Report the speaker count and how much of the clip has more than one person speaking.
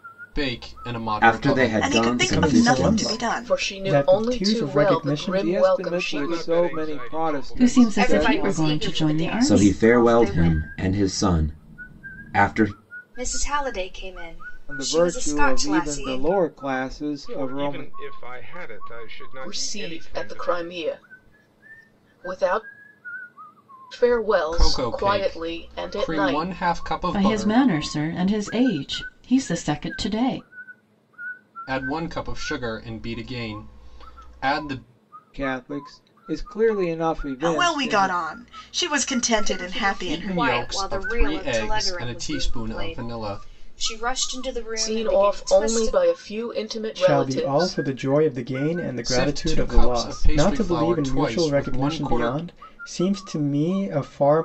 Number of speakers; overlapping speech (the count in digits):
9, about 48%